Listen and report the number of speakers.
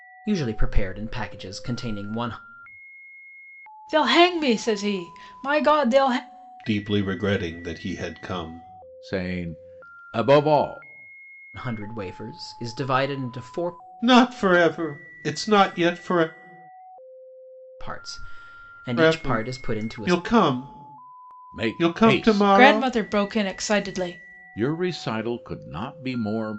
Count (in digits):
4